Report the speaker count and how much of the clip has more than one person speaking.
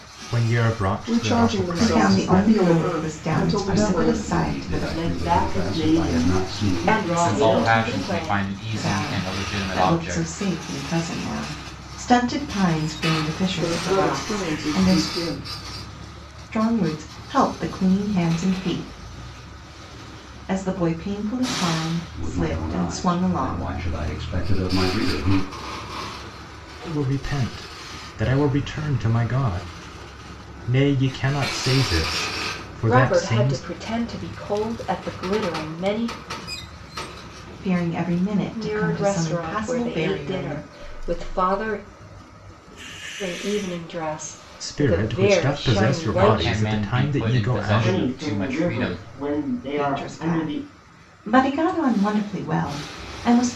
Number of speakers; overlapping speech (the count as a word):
seven, about 38%